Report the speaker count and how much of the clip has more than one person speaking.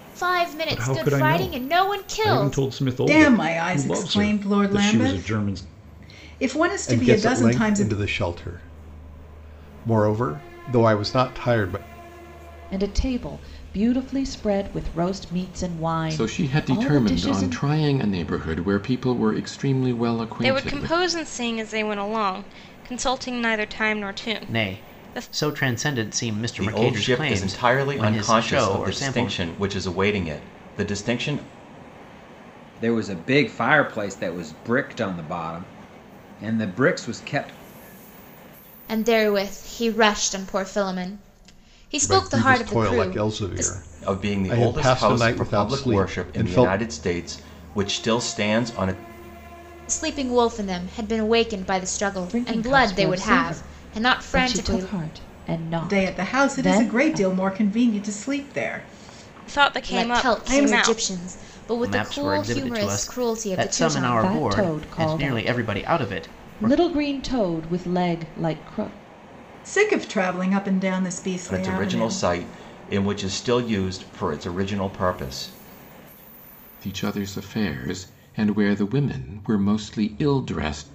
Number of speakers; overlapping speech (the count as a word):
ten, about 34%